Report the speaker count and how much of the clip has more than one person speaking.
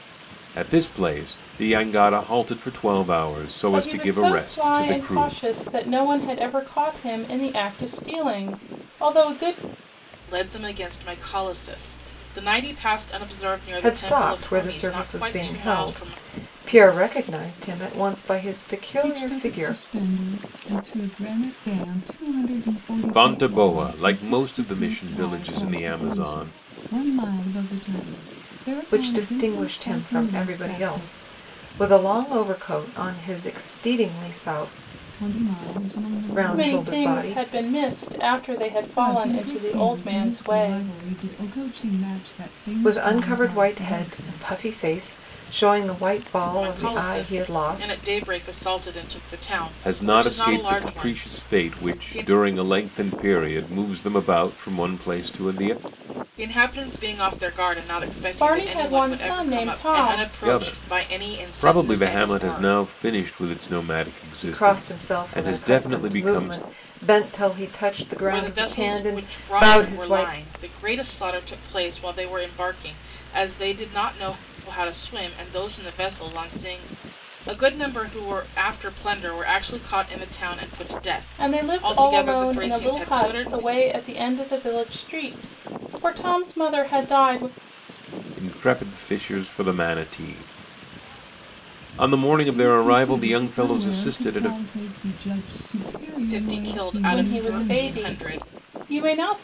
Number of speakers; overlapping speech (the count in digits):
5, about 35%